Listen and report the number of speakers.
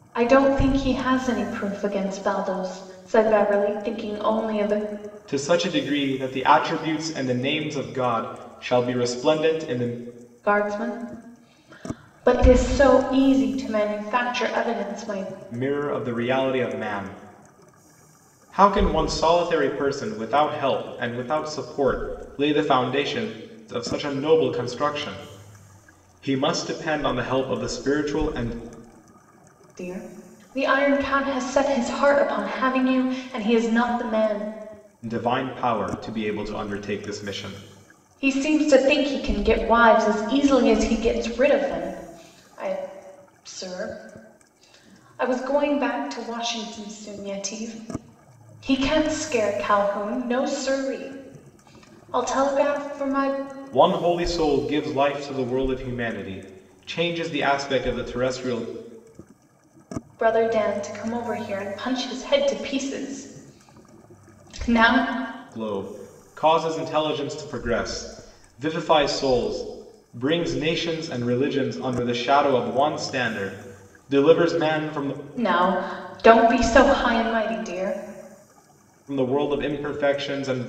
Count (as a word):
two